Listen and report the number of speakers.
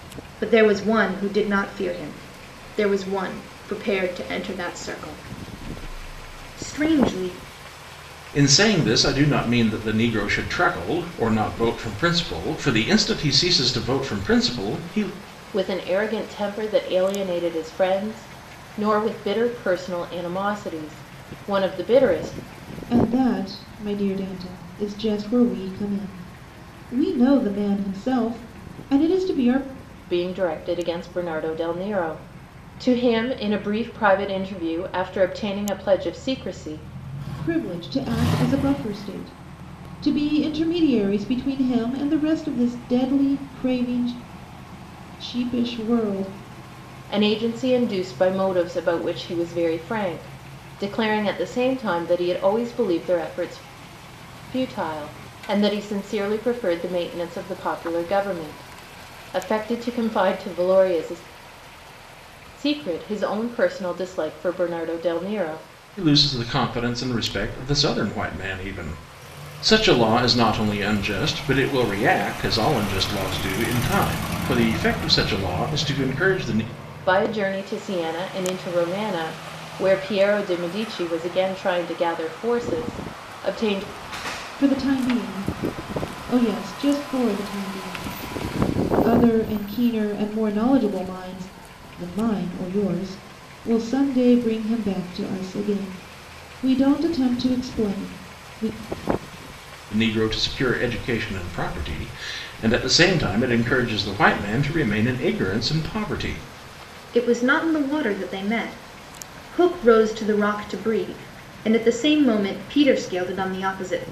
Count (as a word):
four